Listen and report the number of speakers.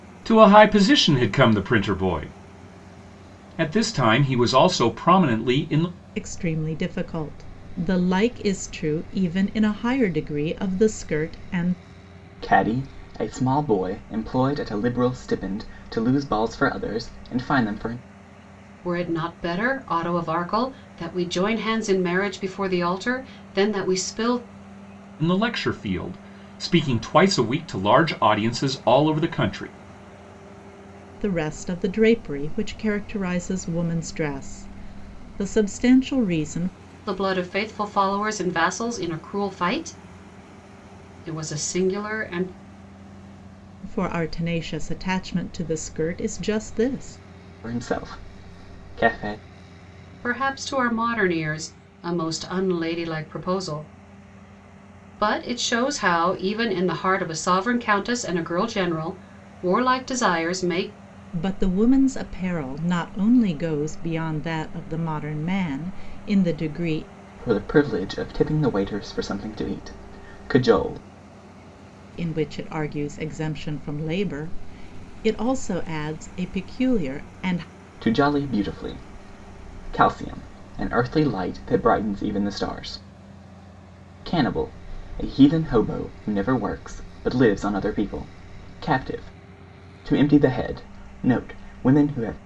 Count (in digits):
4